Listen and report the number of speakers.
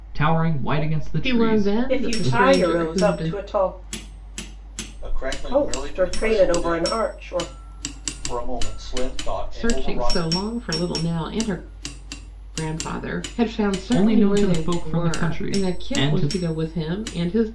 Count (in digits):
4